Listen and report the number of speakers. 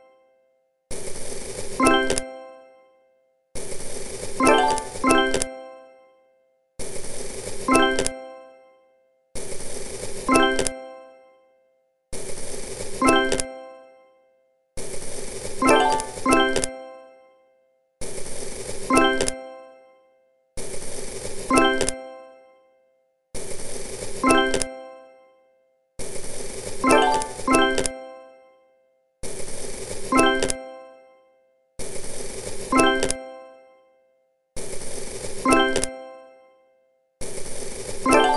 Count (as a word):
zero